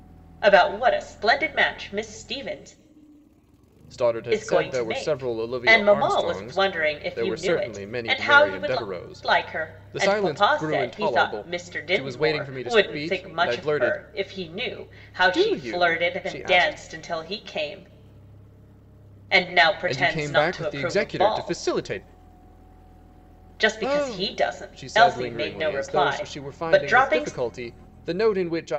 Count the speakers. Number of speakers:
2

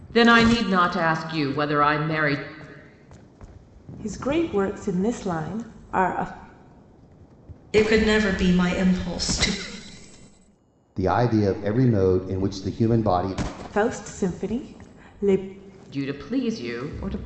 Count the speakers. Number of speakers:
4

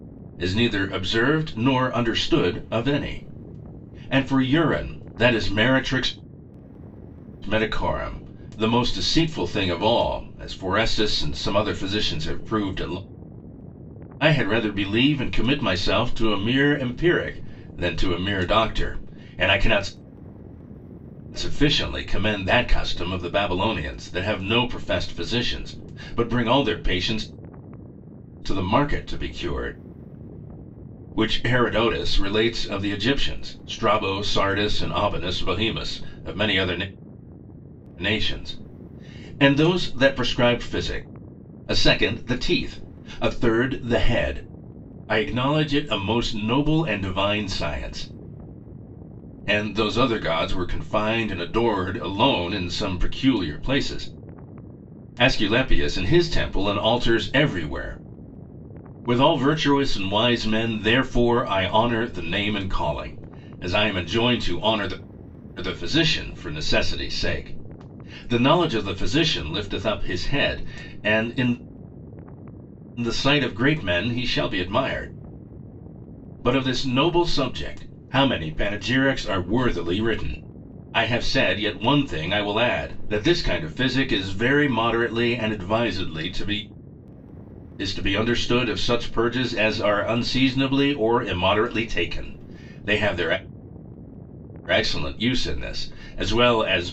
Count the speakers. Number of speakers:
1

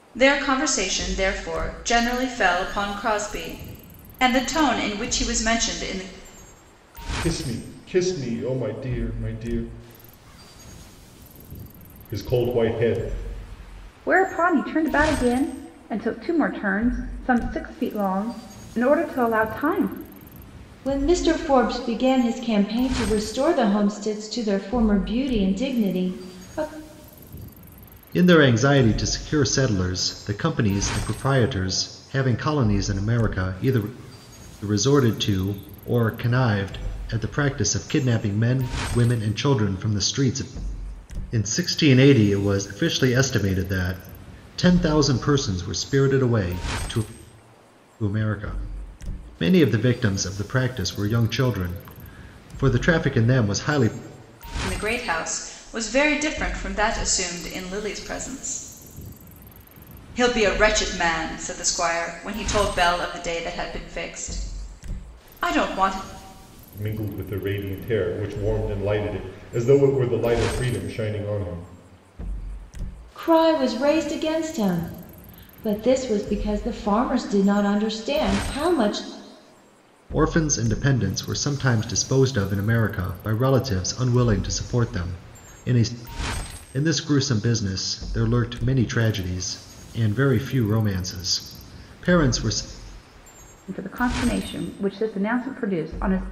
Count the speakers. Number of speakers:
5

